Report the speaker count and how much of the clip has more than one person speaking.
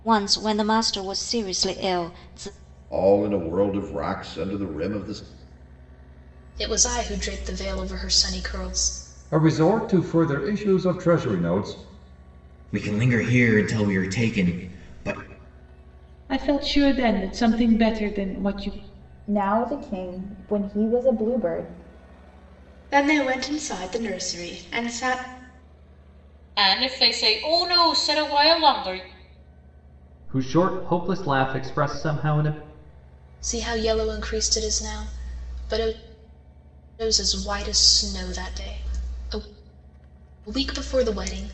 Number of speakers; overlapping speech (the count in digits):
10, no overlap